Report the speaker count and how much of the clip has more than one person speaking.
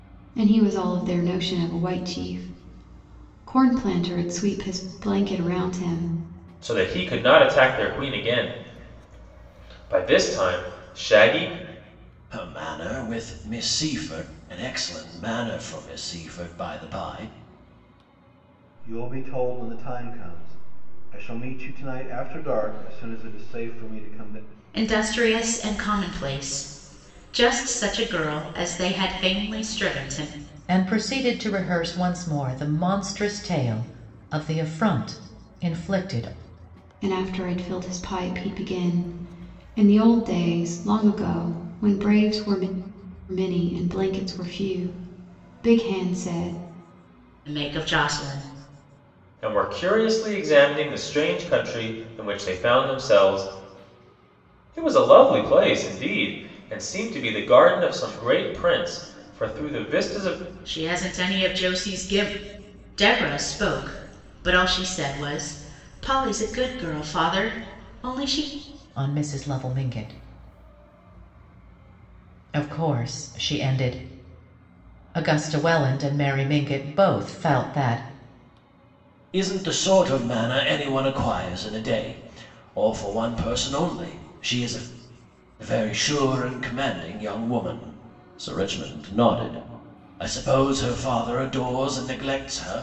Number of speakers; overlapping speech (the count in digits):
6, no overlap